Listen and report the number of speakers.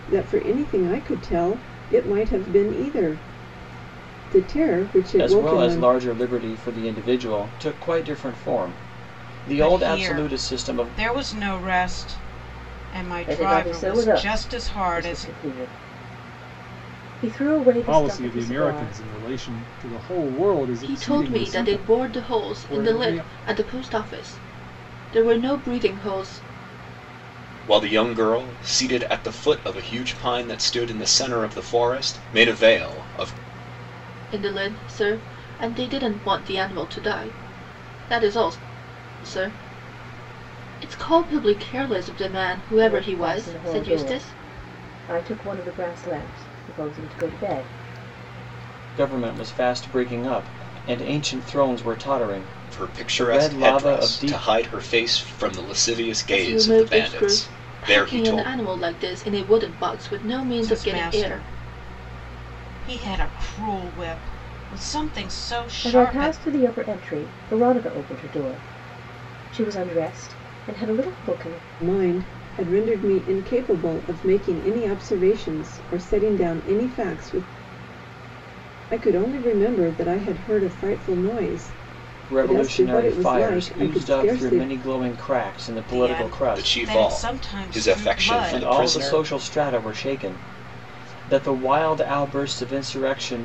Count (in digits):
7